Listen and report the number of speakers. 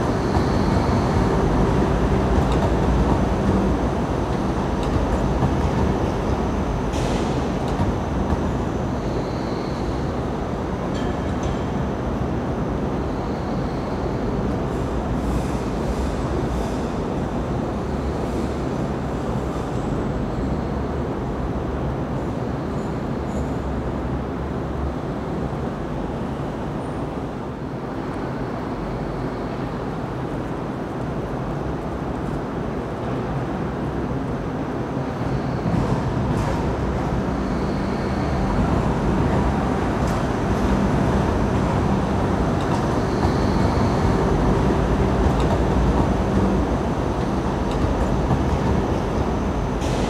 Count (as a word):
zero